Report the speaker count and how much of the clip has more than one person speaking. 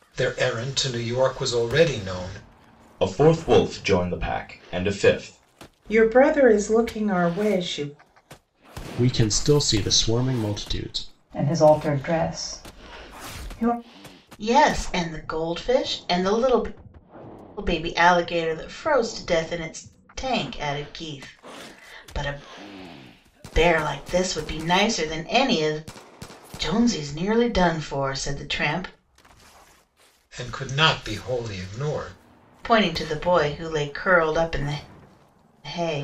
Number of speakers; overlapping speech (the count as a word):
six, no overlap